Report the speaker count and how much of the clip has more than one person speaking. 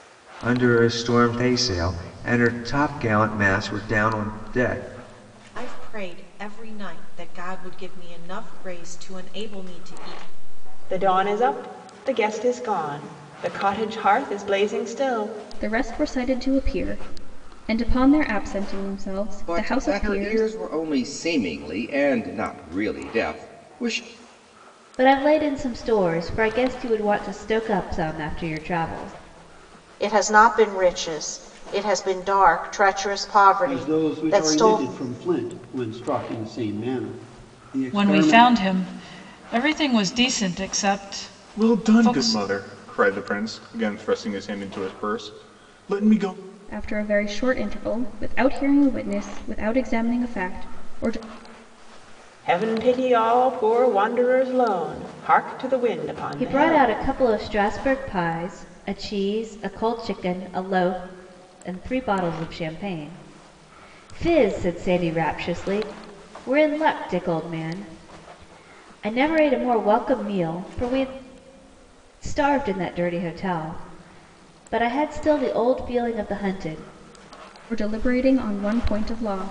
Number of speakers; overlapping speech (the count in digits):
10, about 6%